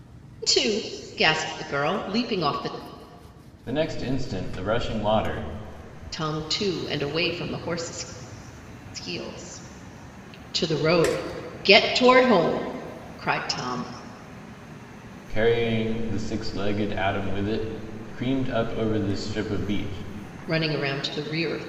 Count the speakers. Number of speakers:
2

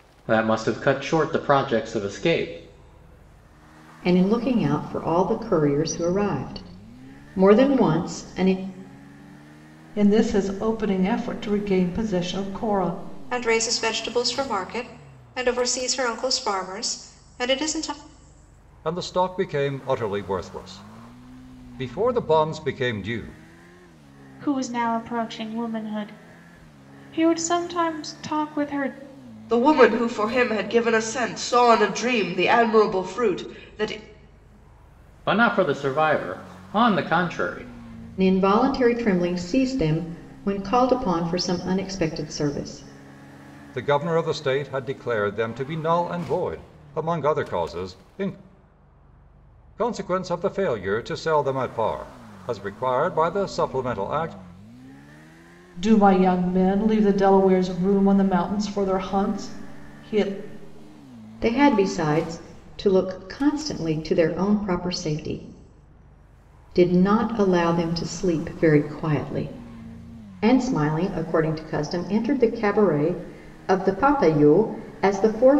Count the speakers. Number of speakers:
7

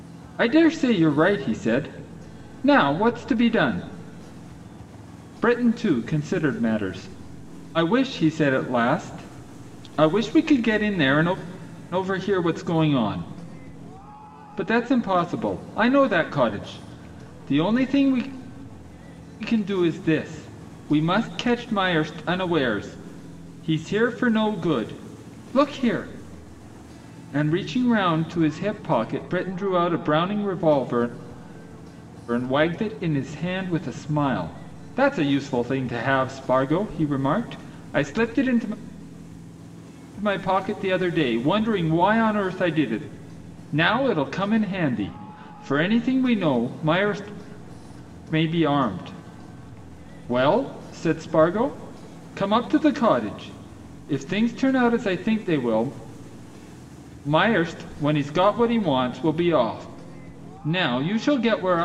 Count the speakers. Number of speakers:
1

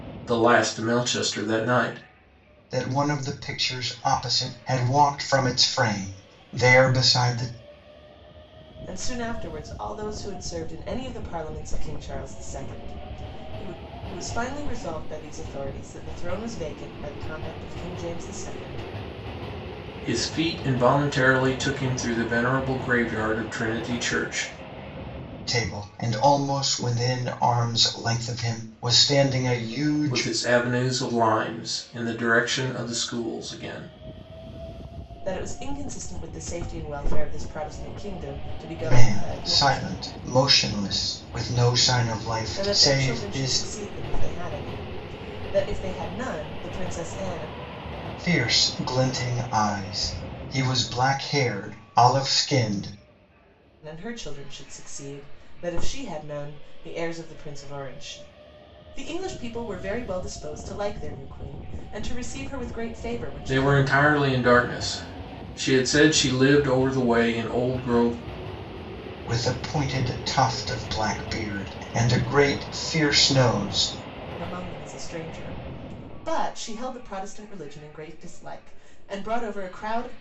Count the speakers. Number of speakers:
3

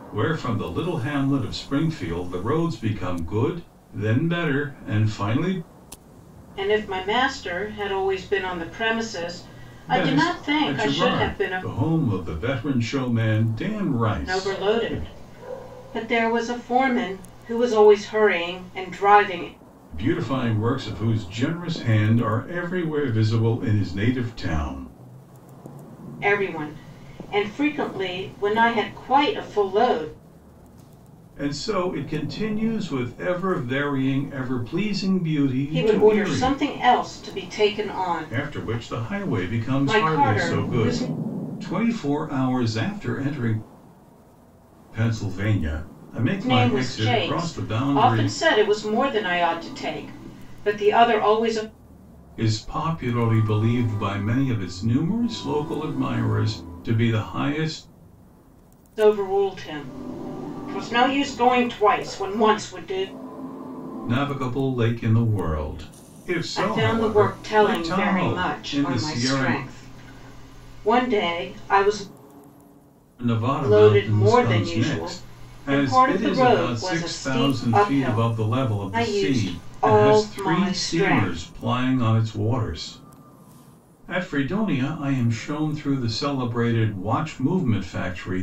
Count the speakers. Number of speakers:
2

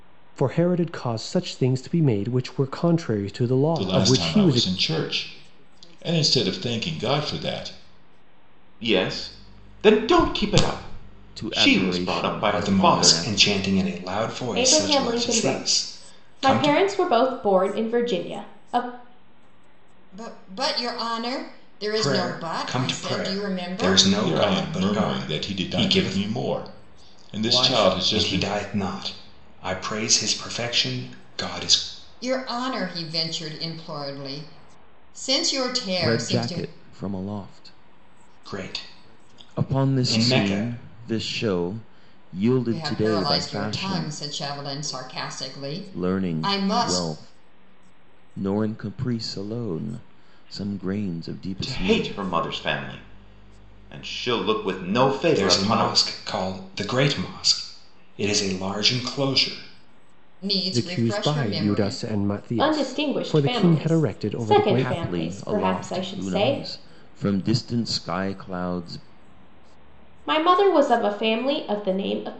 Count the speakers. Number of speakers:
7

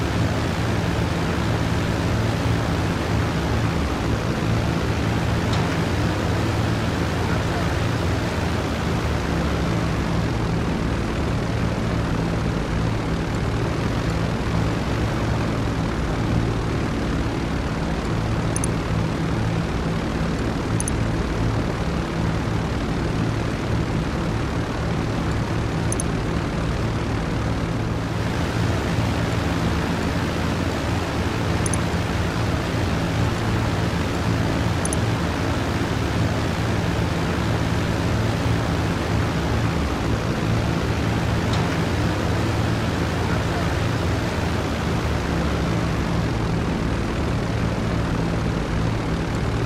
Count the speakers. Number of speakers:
0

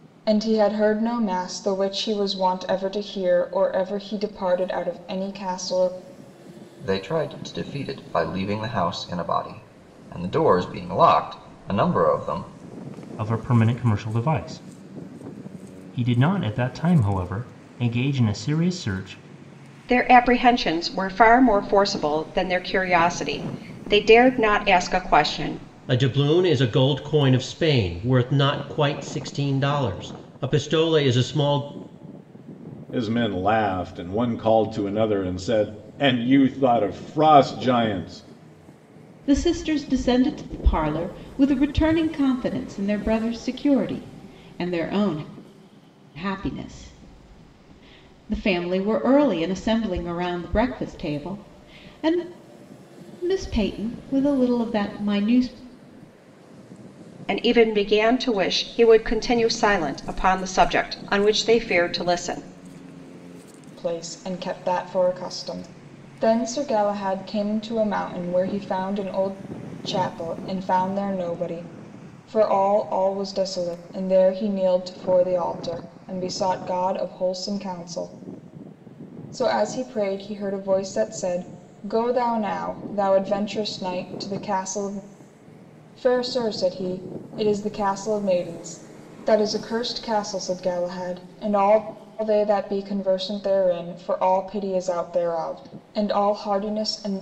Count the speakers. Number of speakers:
7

